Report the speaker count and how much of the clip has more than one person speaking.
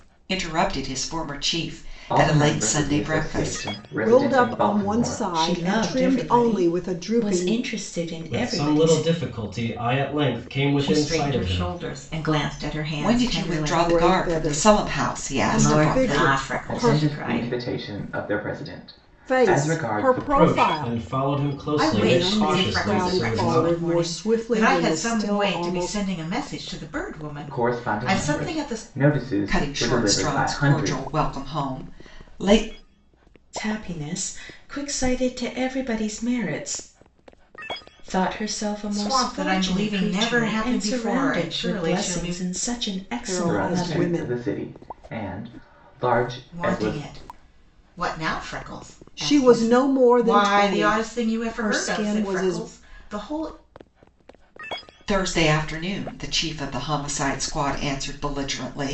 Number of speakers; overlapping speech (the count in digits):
6, about 51%